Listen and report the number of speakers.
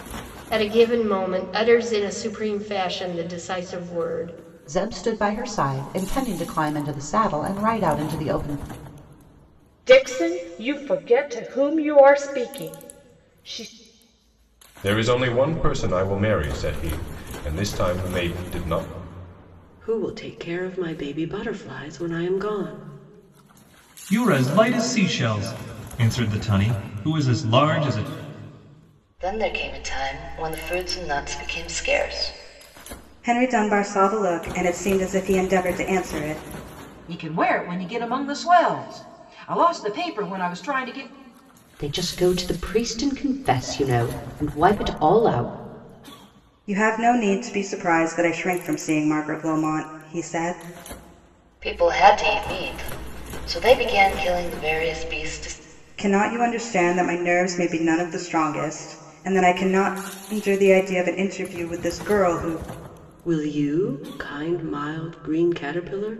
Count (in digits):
10